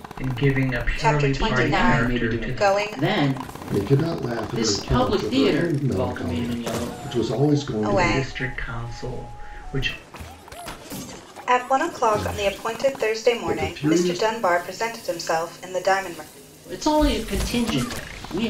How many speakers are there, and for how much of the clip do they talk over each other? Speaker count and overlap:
four, about 39%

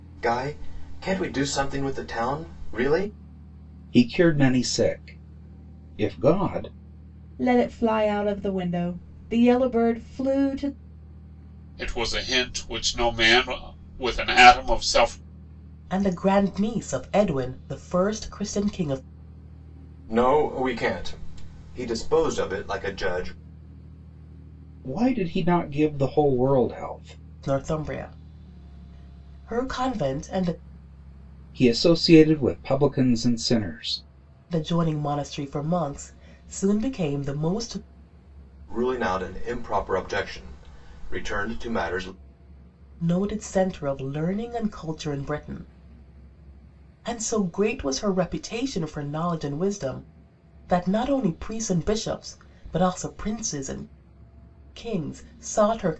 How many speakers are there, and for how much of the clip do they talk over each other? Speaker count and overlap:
five, no overlap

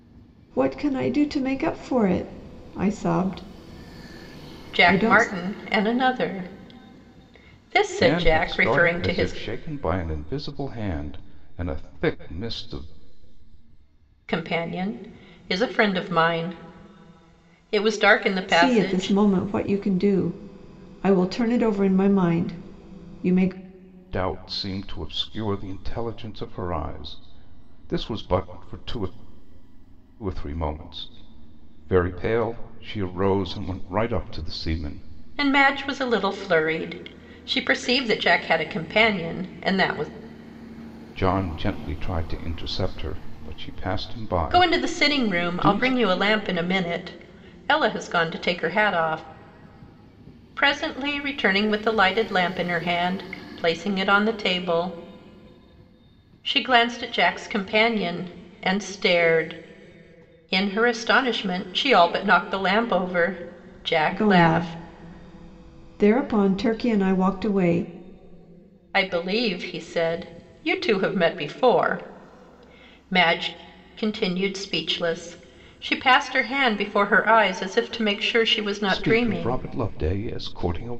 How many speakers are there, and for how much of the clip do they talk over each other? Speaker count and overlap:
three, about 7%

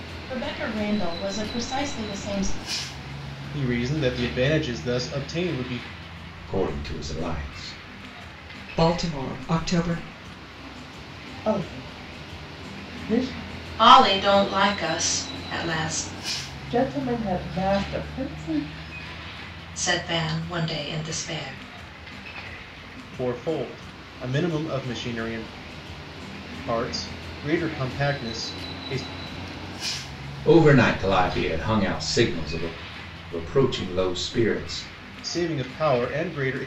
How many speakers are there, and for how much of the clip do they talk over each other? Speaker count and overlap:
six, no overlap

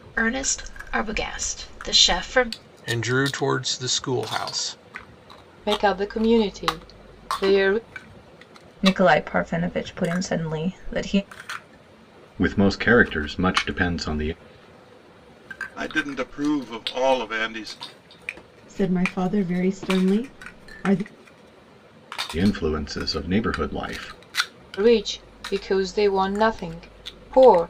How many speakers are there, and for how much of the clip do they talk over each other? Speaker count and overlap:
seven, no overlap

